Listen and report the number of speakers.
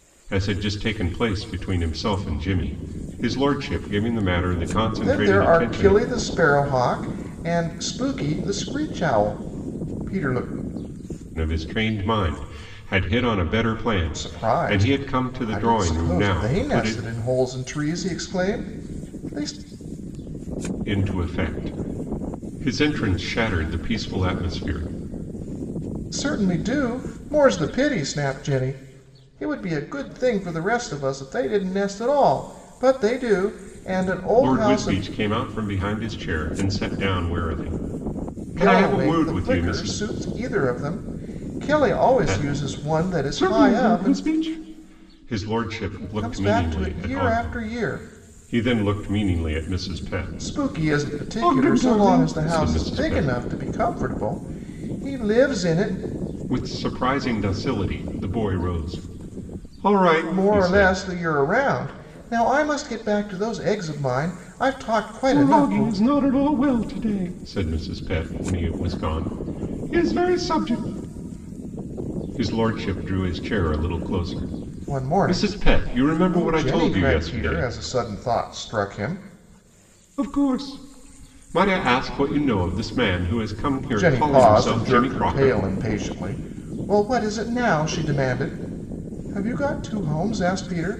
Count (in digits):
2